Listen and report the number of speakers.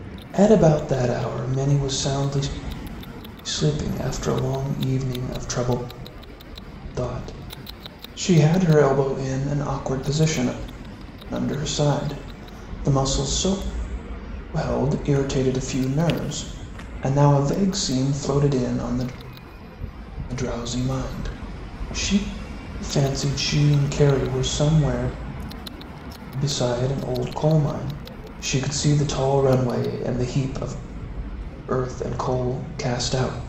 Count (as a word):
one